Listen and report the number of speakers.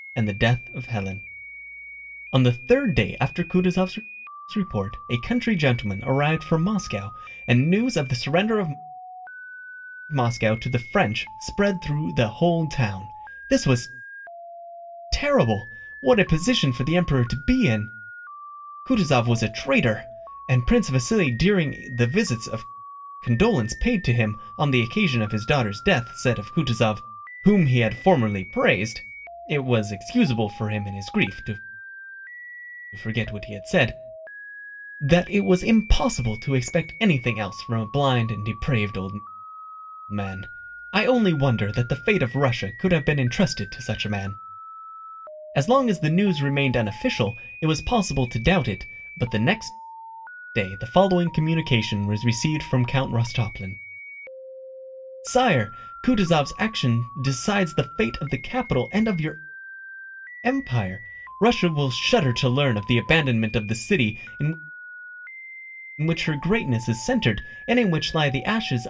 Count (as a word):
one